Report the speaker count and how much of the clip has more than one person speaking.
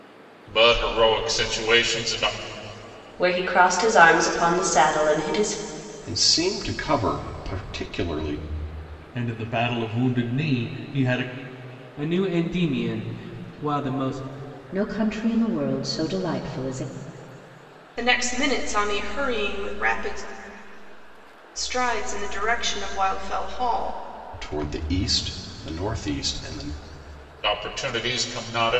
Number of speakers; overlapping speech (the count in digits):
7, no overlap